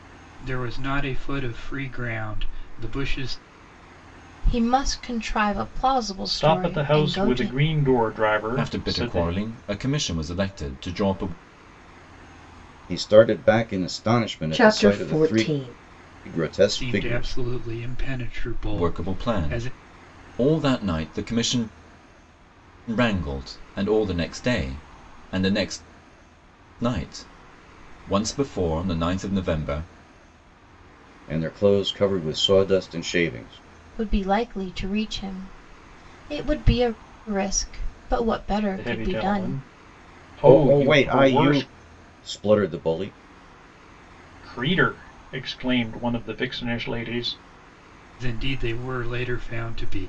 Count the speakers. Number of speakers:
6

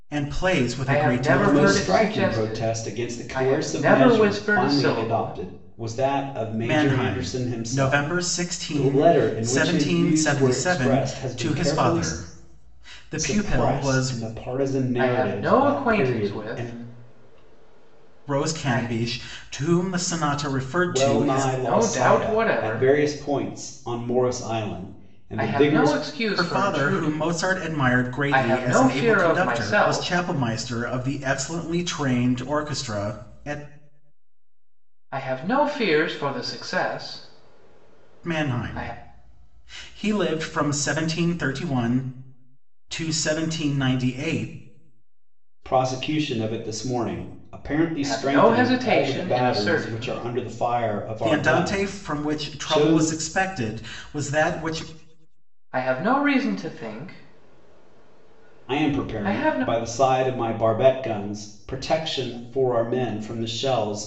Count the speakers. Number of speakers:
3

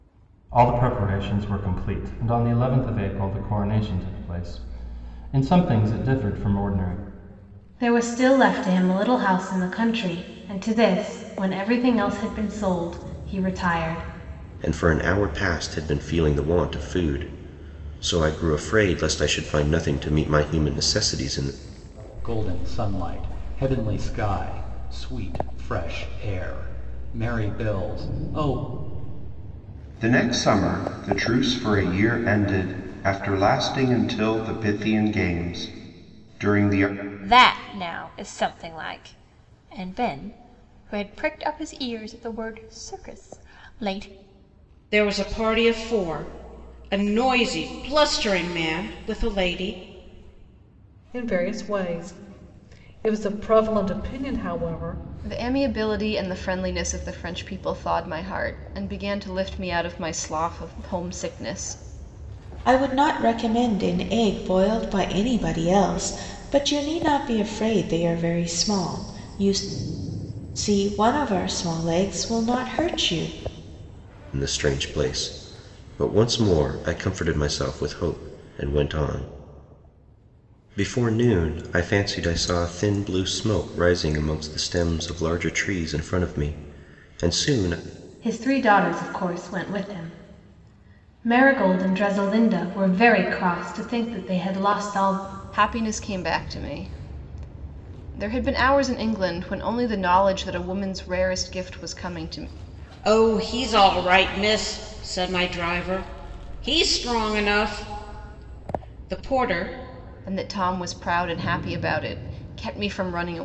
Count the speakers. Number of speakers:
10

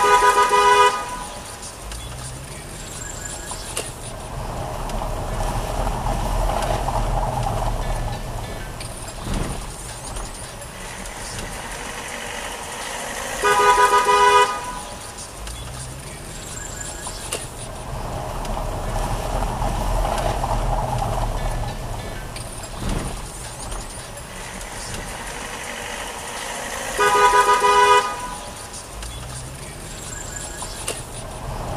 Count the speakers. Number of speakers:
0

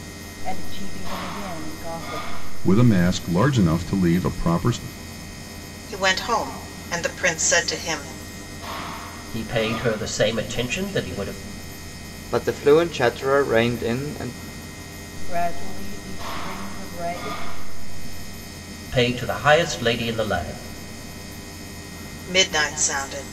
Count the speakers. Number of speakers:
5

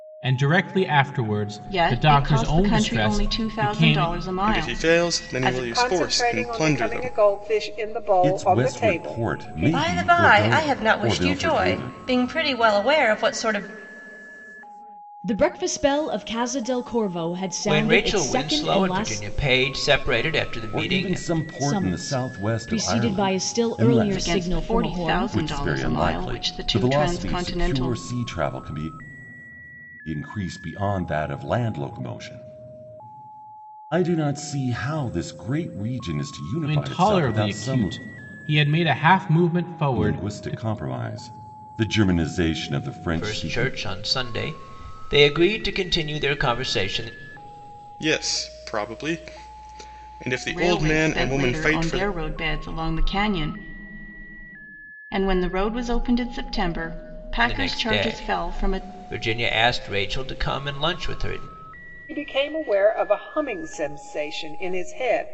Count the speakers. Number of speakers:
8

